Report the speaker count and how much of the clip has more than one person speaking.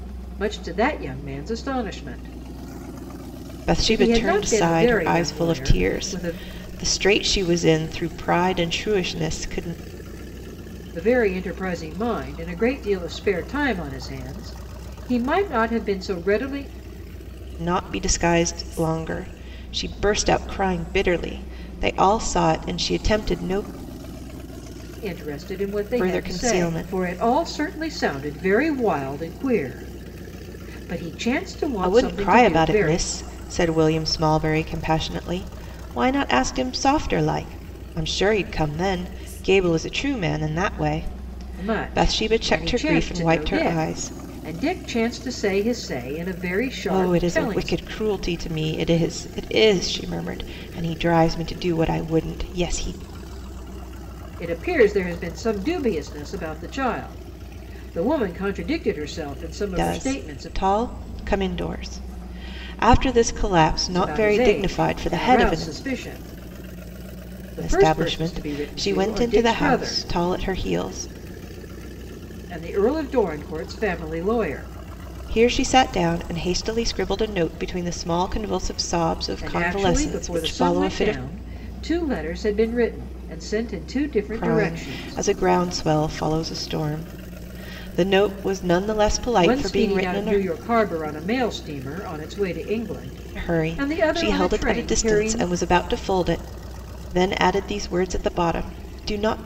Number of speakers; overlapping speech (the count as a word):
two, about 20%